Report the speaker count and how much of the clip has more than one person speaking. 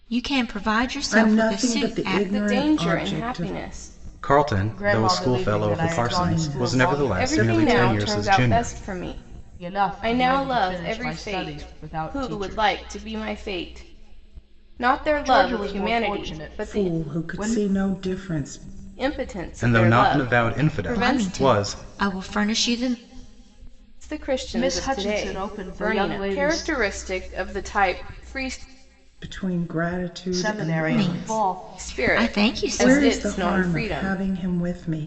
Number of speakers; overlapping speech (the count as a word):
five, about 56%